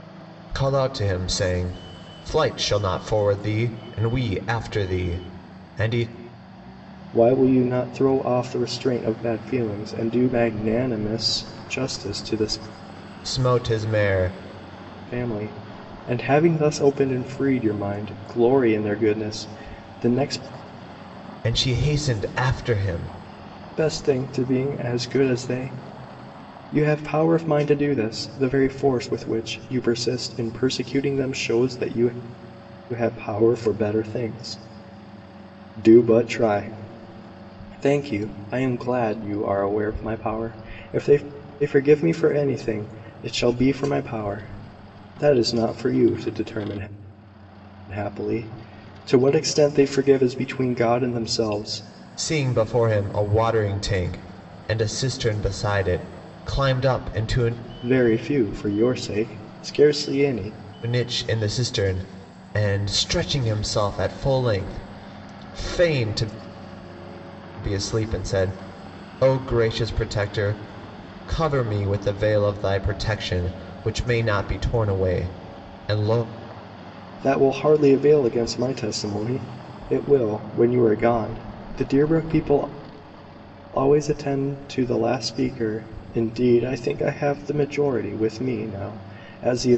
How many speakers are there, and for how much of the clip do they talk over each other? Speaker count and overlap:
two, no overlap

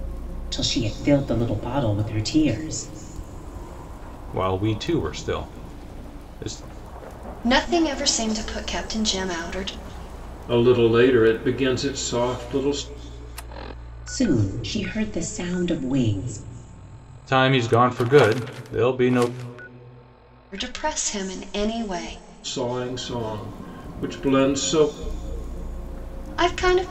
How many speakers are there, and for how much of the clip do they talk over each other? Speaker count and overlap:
four, no overlap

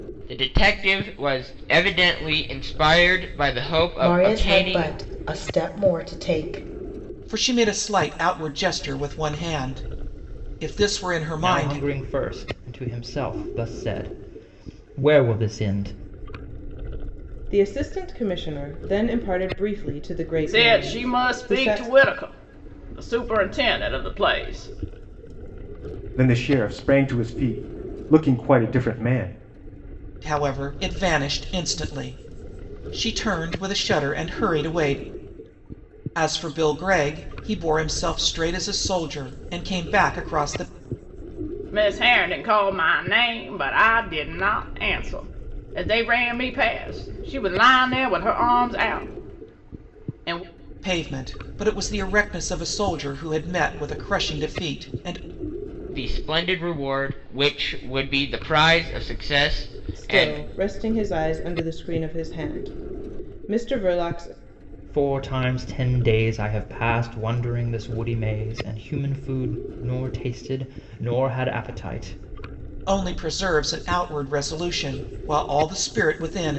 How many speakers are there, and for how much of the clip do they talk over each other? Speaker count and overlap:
seven, about 4%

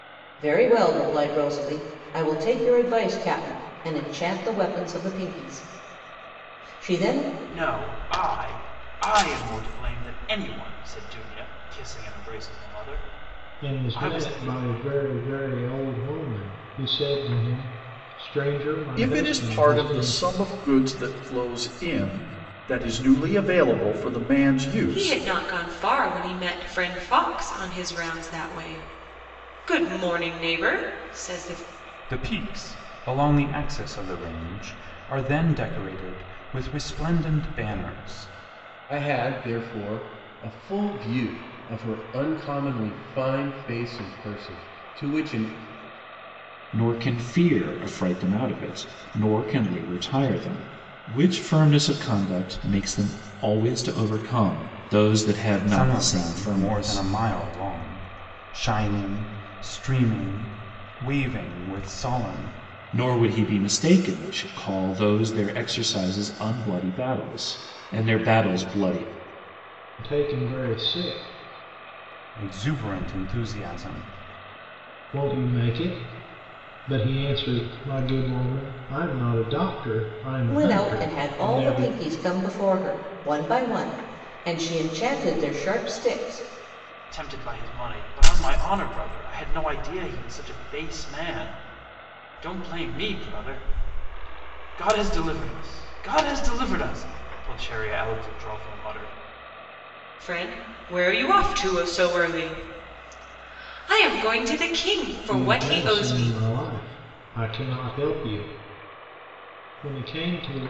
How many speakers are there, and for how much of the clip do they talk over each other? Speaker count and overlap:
eight, about 6%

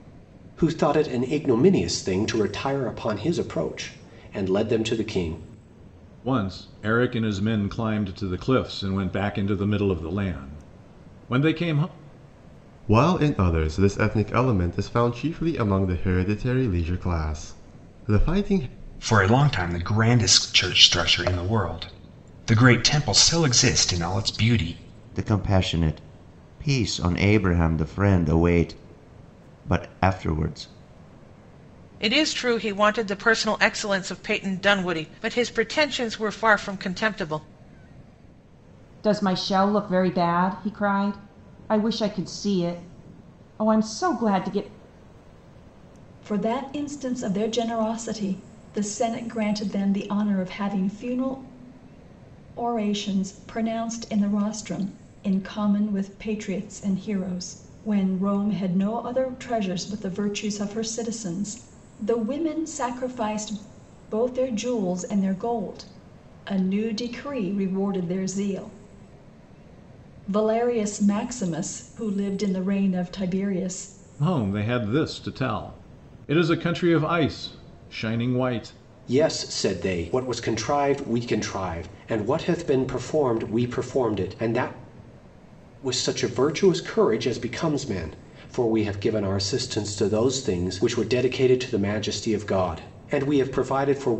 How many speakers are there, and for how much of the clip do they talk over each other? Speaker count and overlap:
eight, no overlap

